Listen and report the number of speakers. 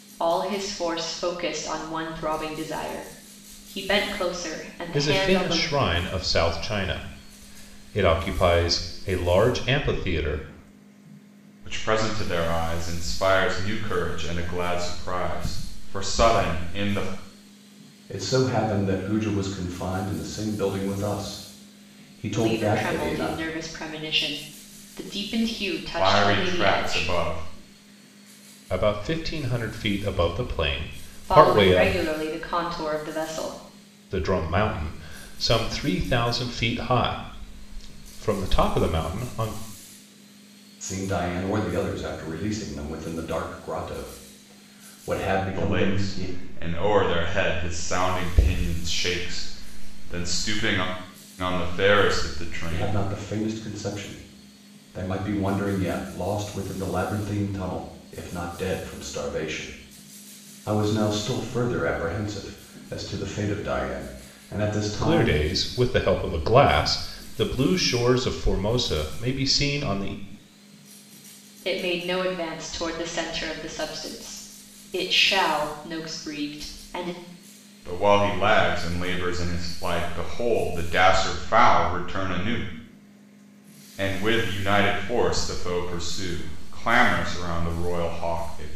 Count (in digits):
4